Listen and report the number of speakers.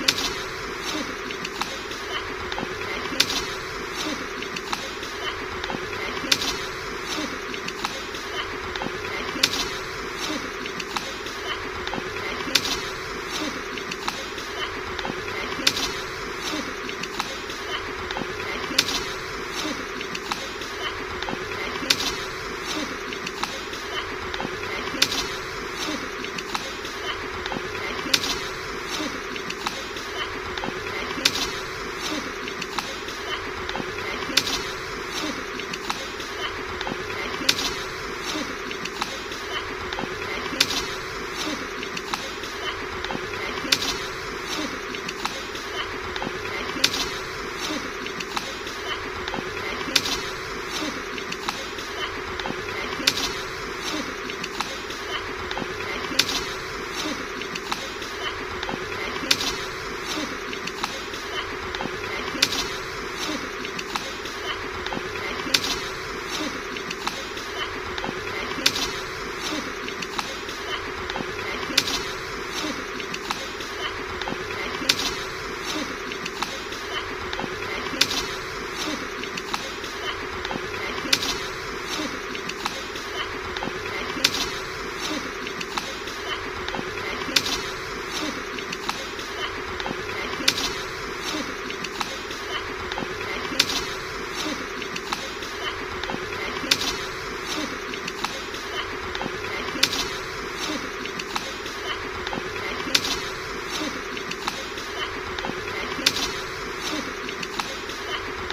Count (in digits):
0